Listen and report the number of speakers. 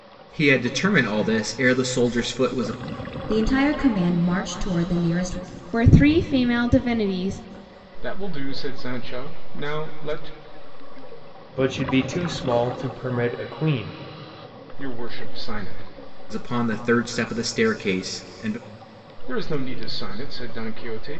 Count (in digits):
5